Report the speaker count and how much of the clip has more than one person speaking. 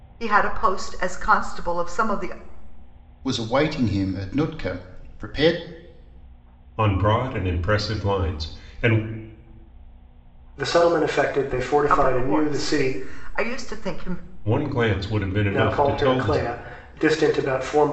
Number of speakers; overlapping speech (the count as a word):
four, about 11%